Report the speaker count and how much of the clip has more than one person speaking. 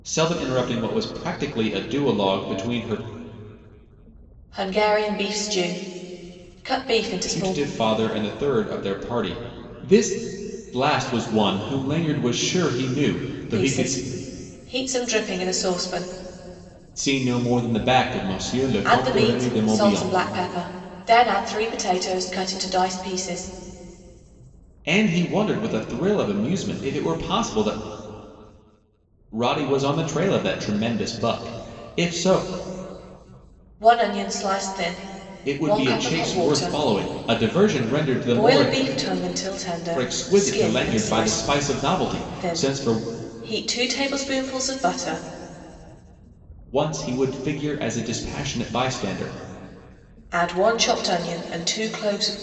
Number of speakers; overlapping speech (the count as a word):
two, about 12%